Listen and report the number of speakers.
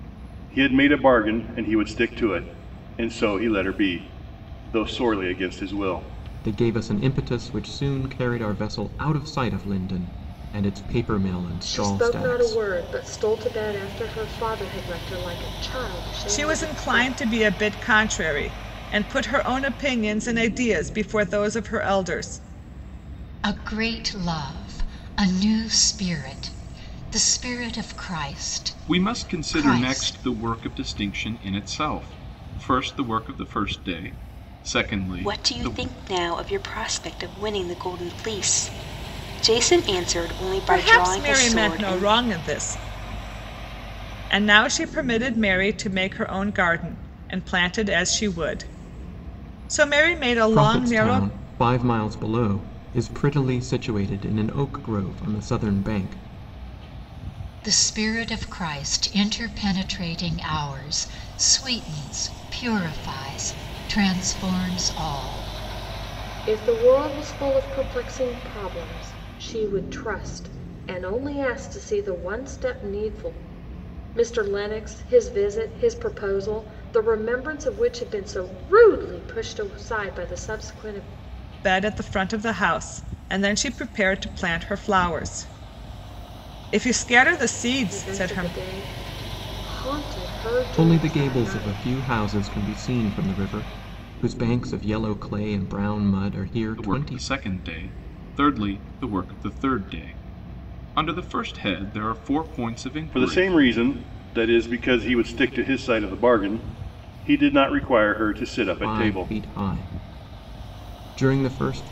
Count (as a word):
seven